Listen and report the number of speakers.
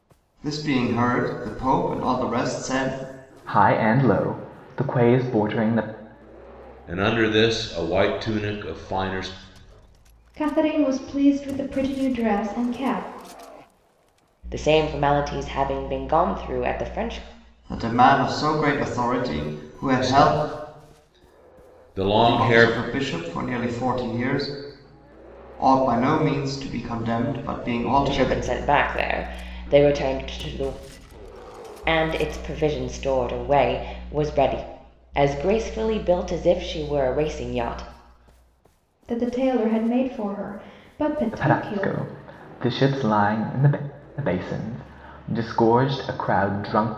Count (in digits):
5